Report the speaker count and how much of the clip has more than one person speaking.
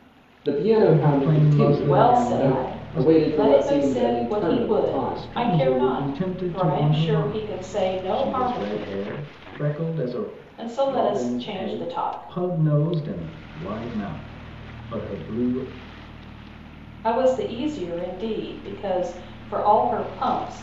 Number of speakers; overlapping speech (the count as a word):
three, about 43%